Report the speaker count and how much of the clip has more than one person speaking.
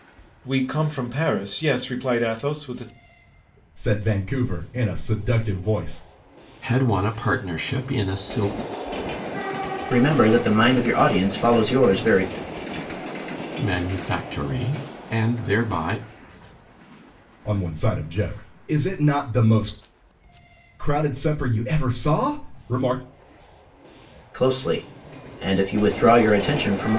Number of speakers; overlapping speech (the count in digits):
4, no overlap